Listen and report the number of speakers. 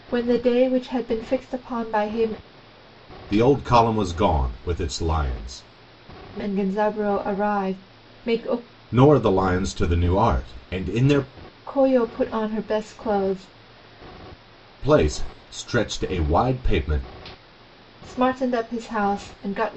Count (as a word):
two